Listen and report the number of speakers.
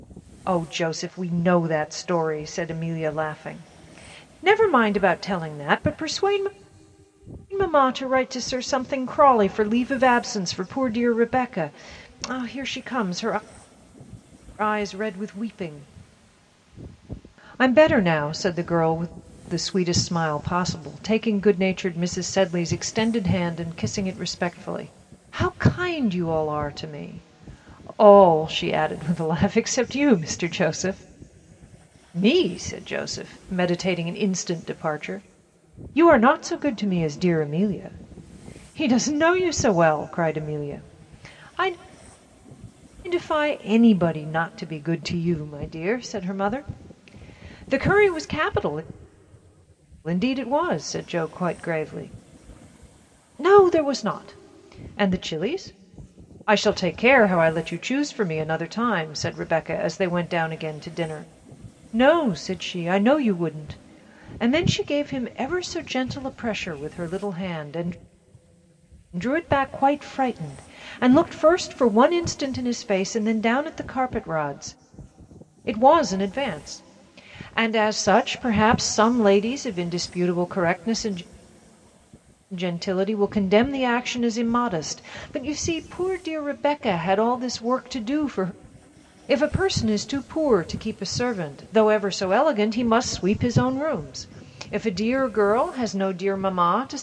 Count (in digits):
1